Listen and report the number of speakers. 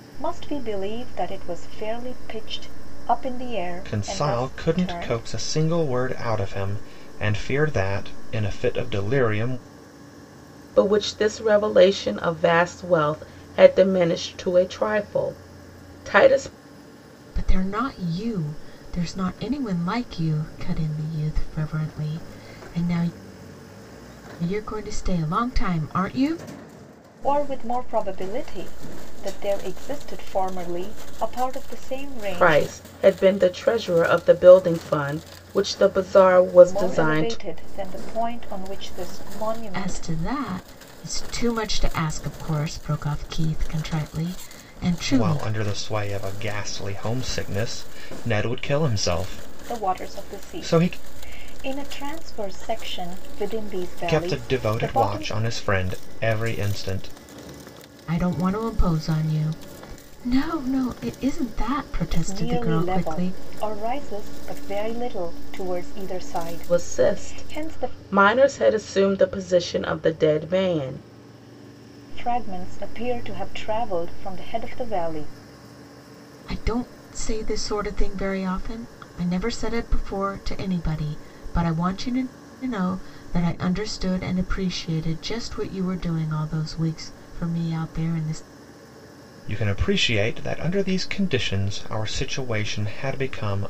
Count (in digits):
4